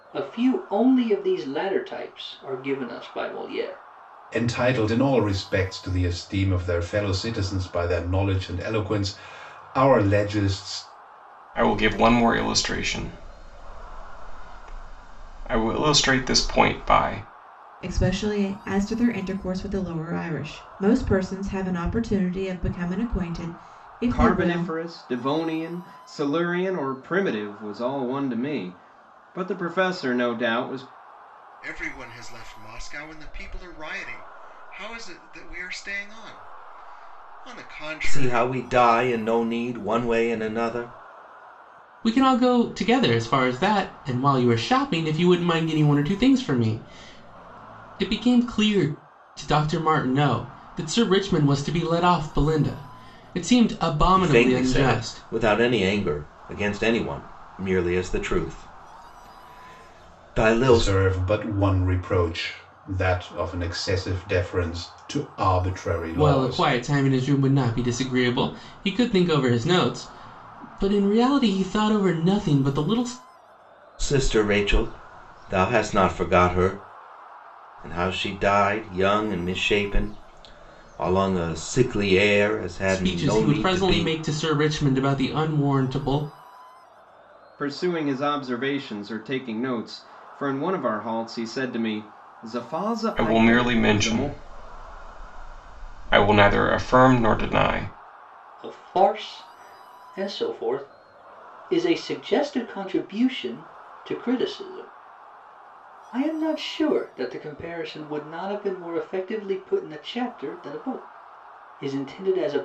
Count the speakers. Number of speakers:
8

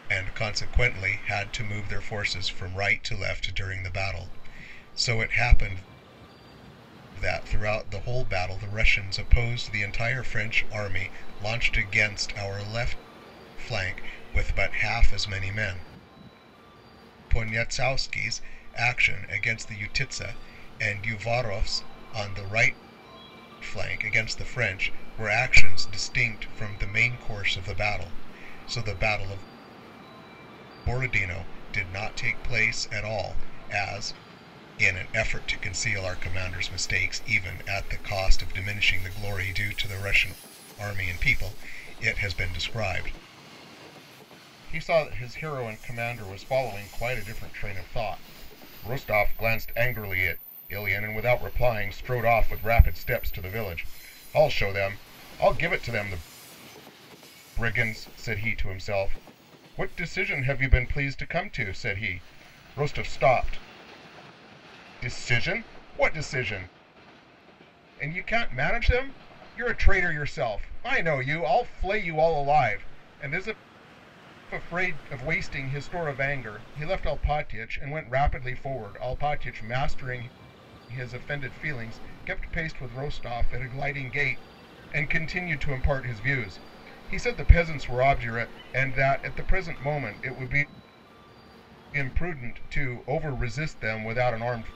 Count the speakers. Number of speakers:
1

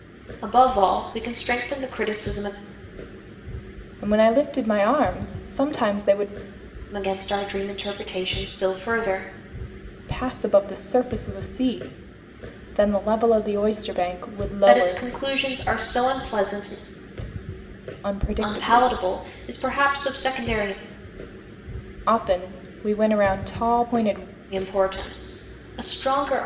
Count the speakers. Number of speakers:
2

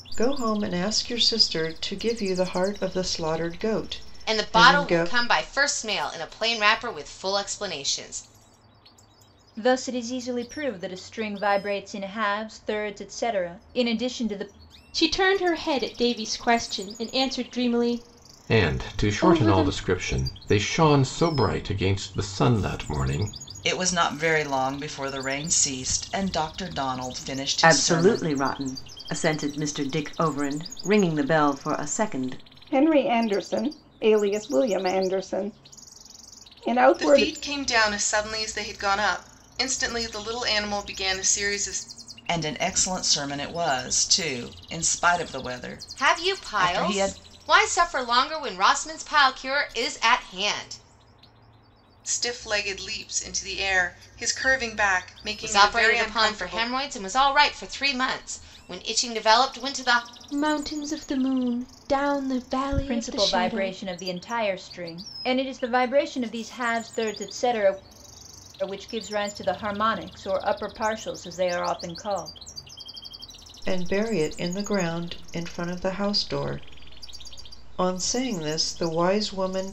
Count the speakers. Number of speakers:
9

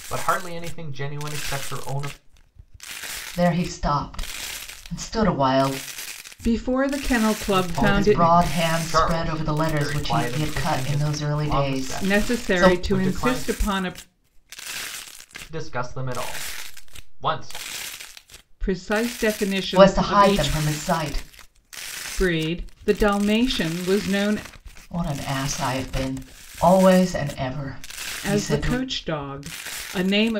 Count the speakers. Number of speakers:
3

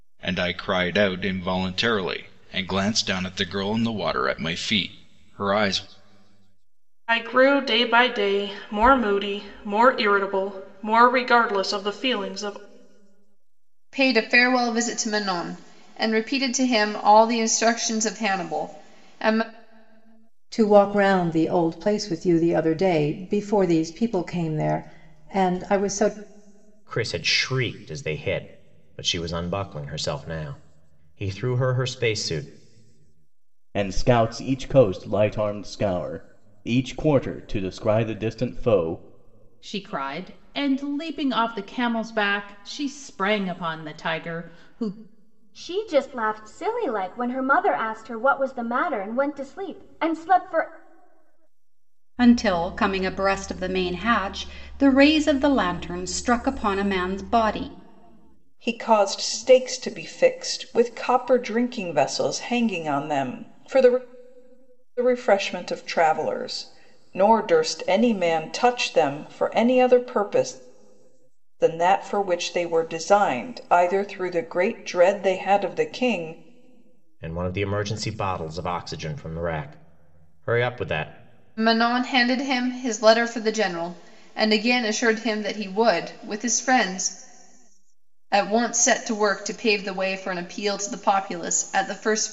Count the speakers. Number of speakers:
10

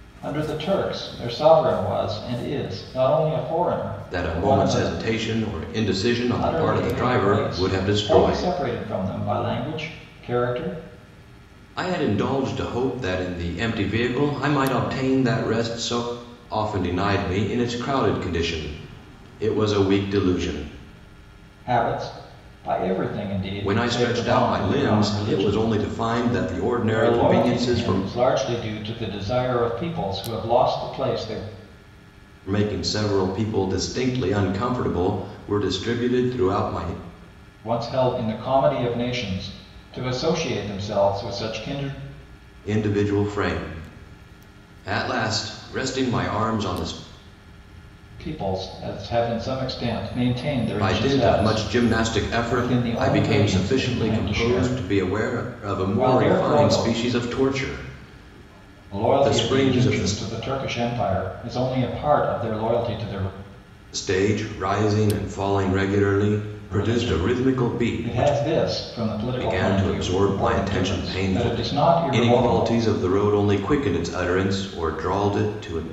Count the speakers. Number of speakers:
2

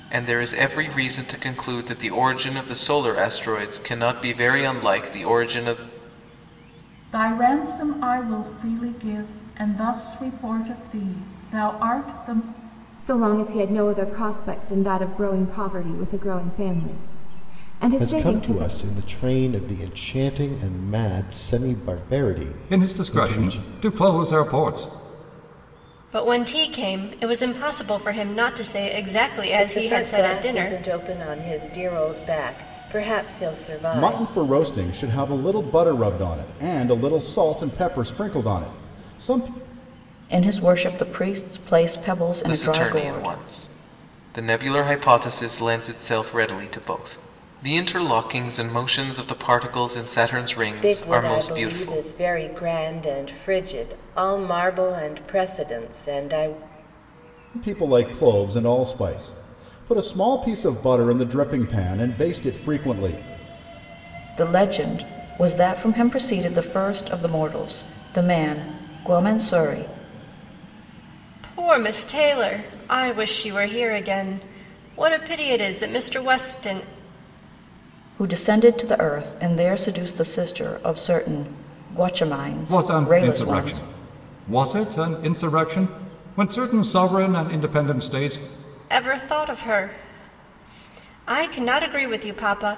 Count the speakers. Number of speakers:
9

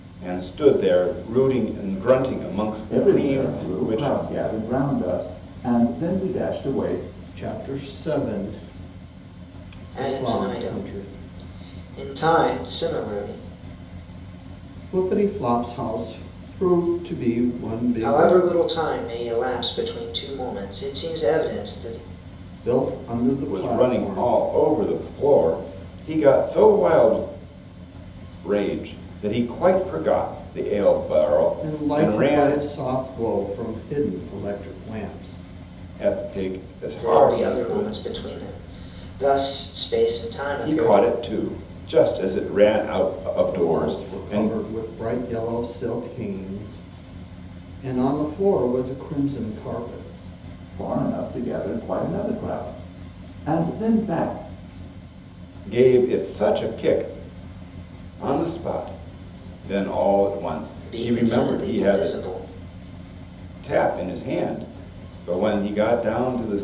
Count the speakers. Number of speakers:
4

